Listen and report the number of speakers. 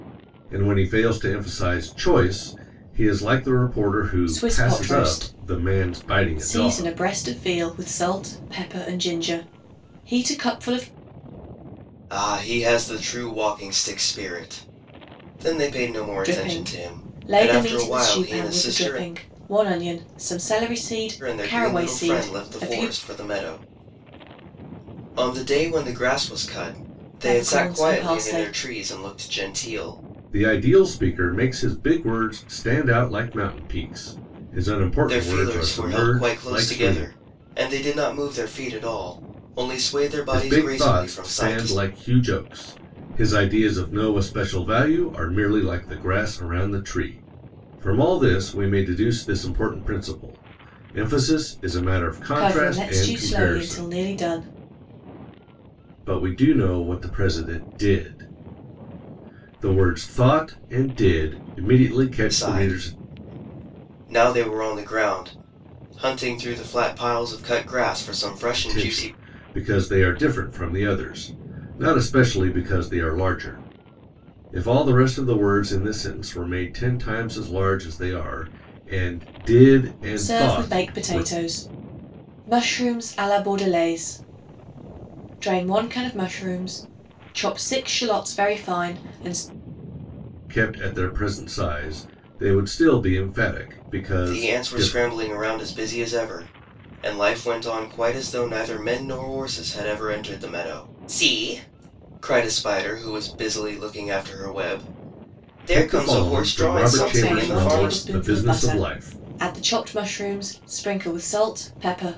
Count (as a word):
three